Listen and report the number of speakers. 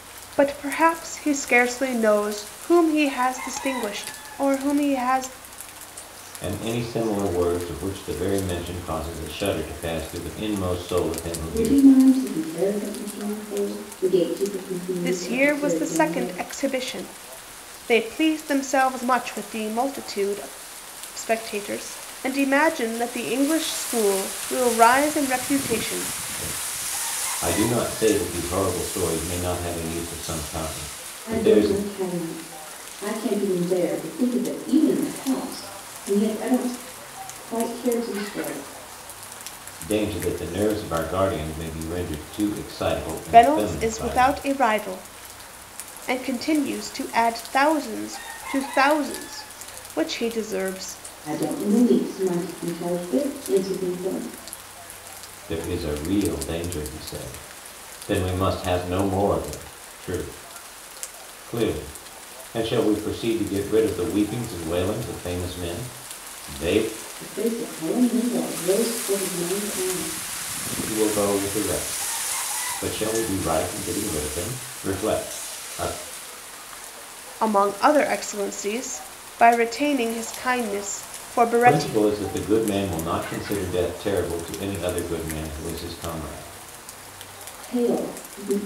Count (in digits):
3